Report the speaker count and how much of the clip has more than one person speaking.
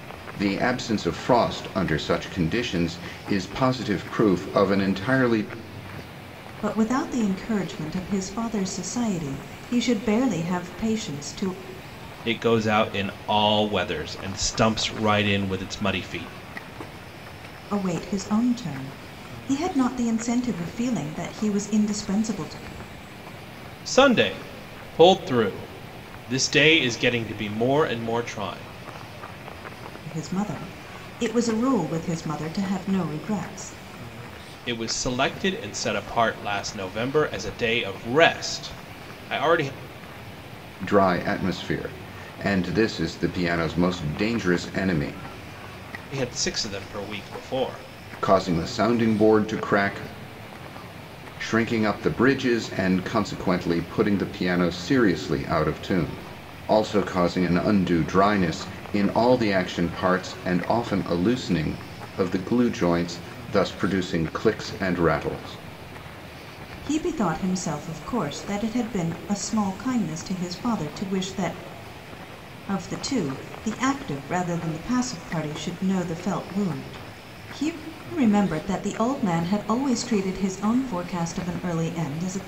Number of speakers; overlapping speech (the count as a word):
three, no overlap